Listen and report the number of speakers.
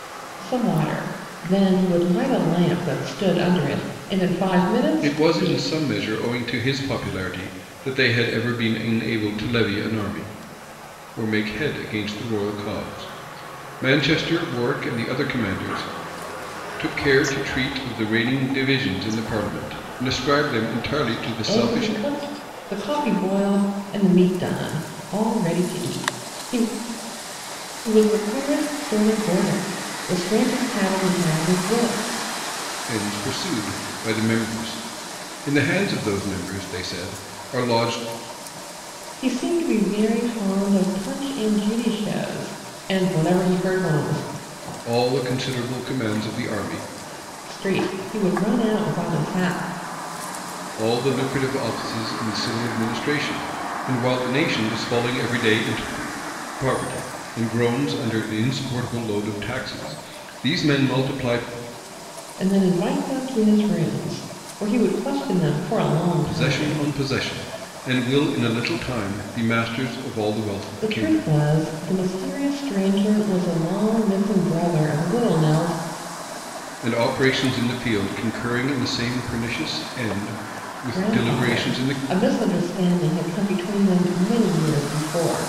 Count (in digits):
2